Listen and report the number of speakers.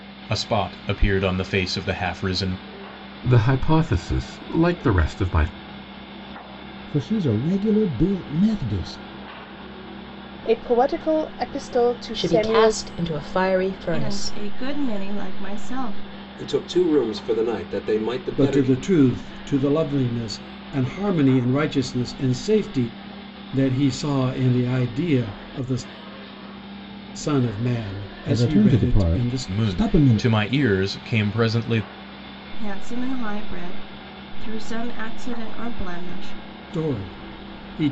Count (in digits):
8